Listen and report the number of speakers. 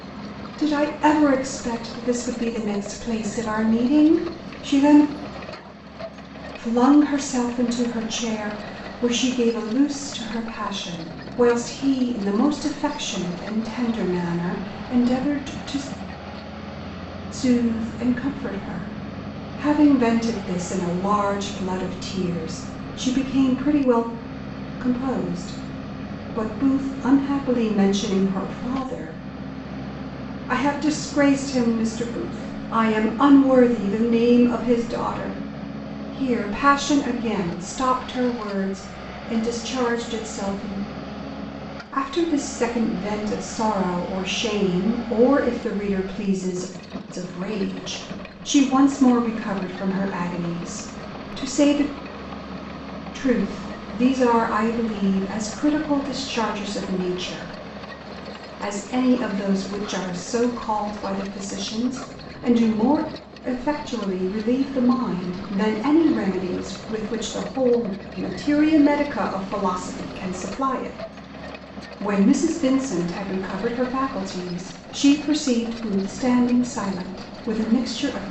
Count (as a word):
one